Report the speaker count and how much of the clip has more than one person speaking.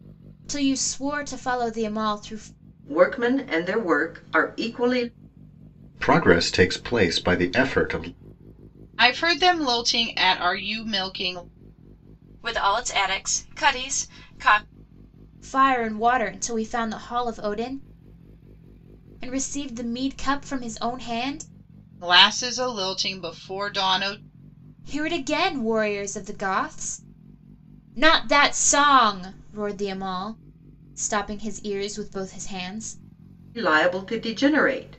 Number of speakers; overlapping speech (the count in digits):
5, no overlap